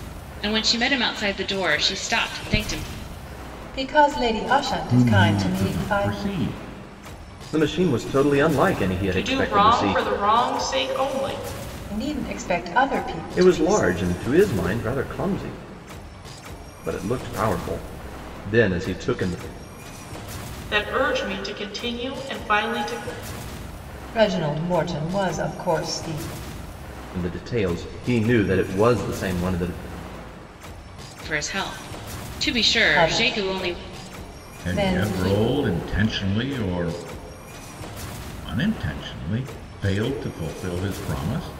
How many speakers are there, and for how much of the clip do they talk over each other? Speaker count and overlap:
5, about 11%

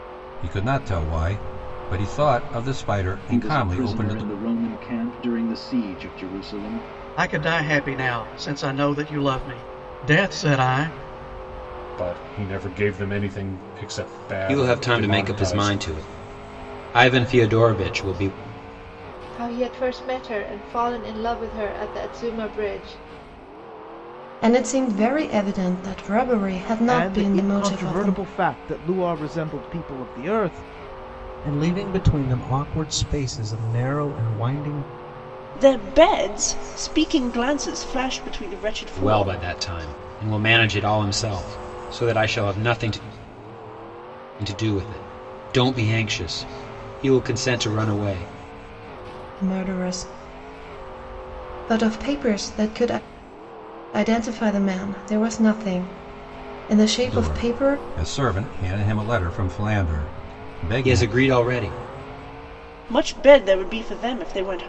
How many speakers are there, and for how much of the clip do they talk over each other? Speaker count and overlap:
10, about 8%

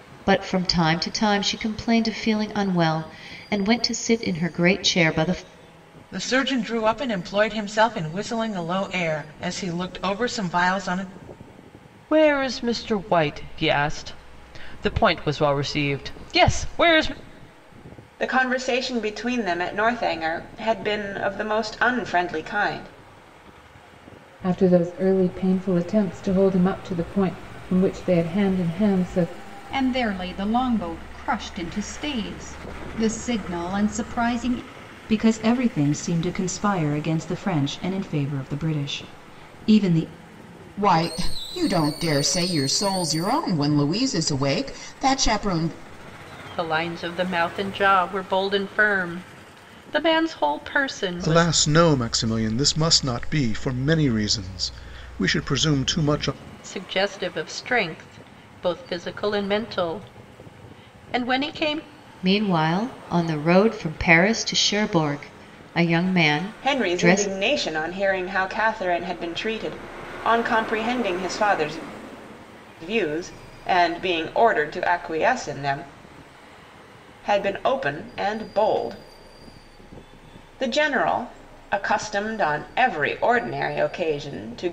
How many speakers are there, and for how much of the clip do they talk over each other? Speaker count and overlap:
10, about 1%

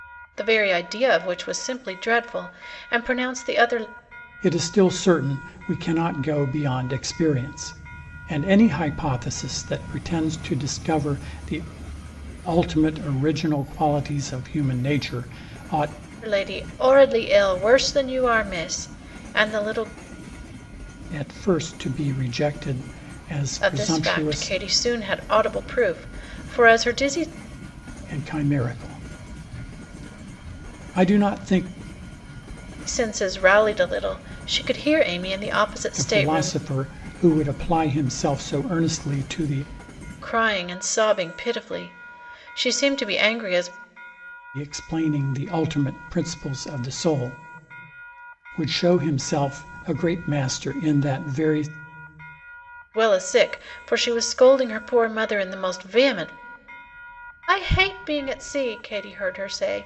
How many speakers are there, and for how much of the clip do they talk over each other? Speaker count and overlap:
2, about 3%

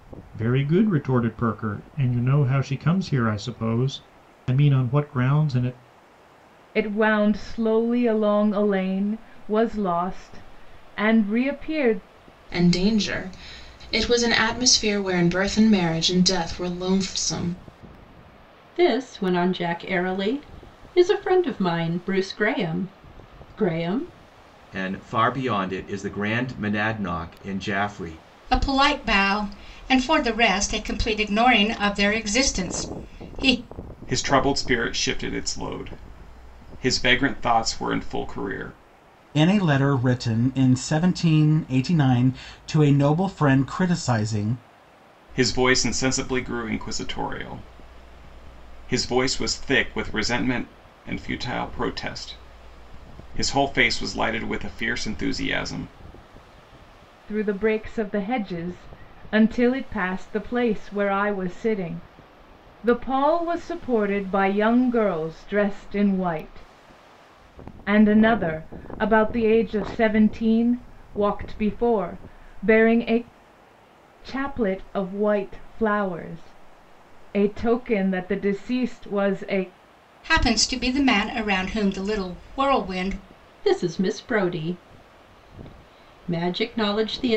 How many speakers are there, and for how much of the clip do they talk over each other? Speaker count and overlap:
8, no overlap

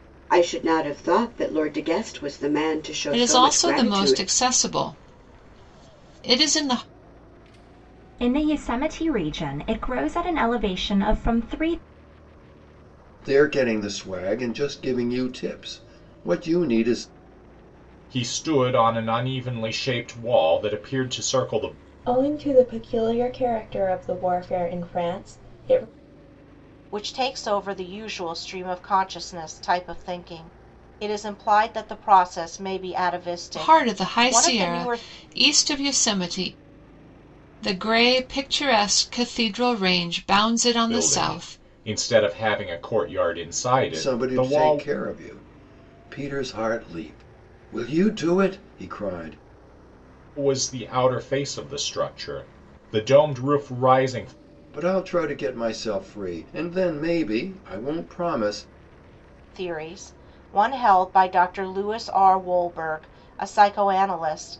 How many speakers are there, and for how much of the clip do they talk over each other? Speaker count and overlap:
7, about 7%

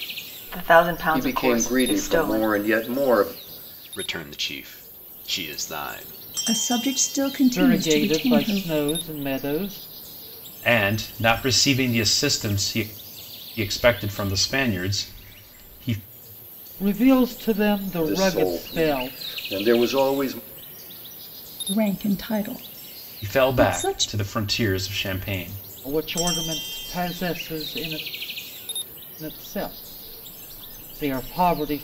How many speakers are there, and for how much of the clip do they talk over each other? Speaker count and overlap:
6, about 15%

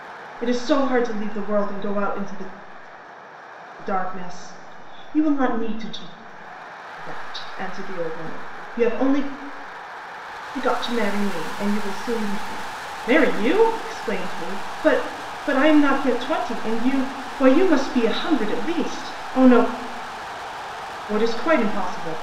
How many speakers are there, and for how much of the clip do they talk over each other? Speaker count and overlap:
1, no overlap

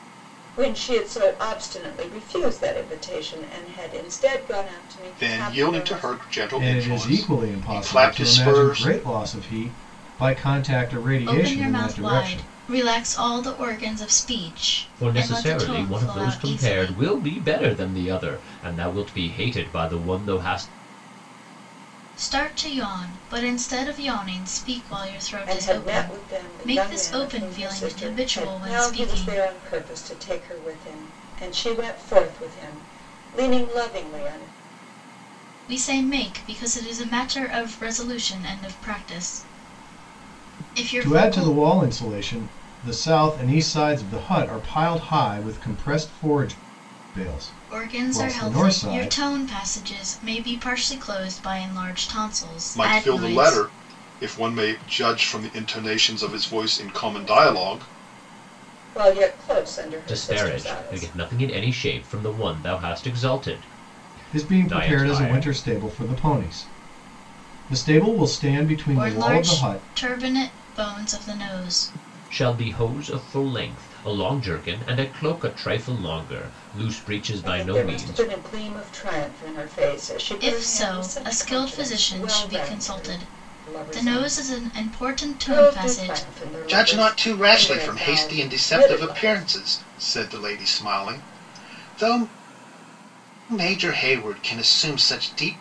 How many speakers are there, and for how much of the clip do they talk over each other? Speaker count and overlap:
5, about 28%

